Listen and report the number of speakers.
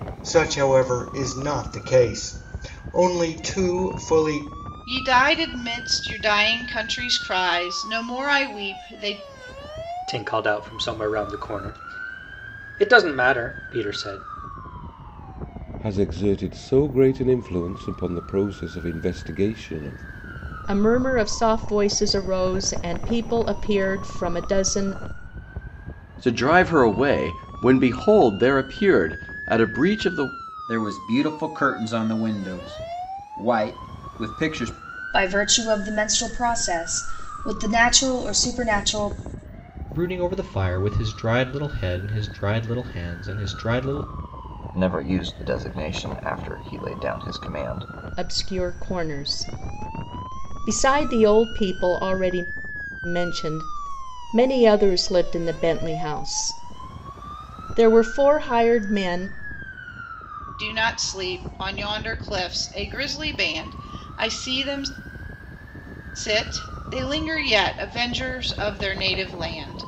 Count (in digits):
10